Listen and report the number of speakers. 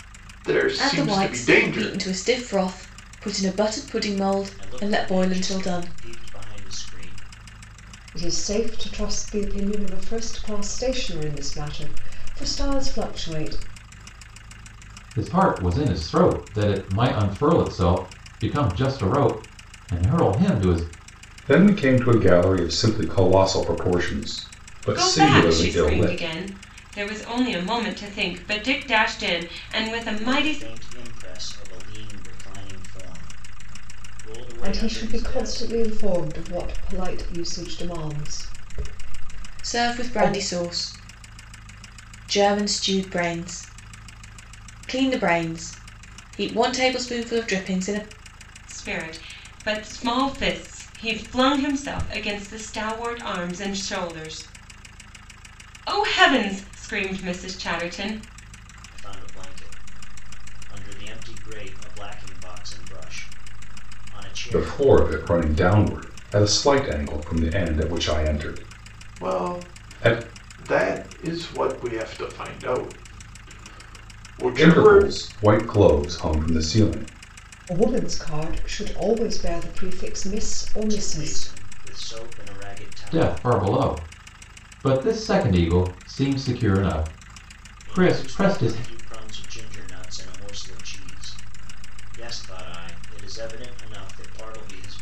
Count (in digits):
7